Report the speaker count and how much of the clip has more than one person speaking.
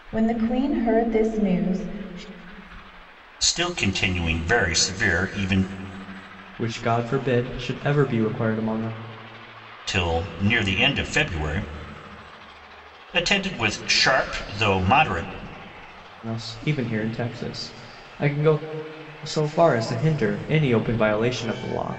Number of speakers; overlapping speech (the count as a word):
three, no overlap